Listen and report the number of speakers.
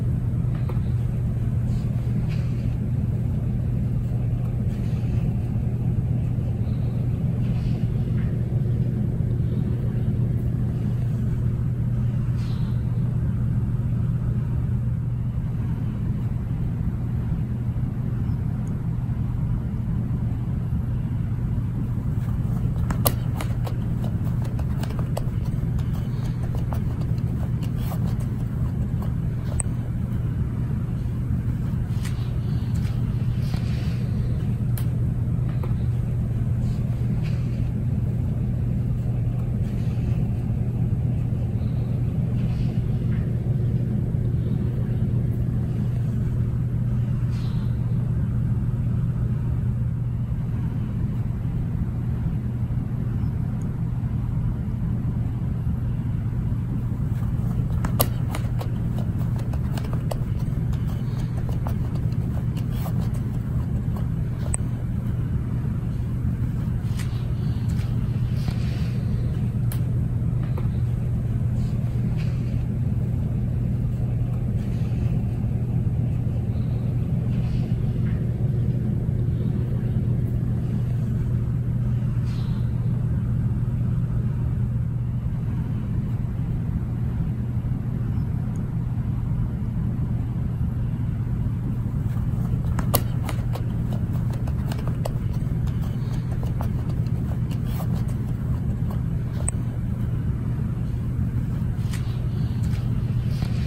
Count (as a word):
zero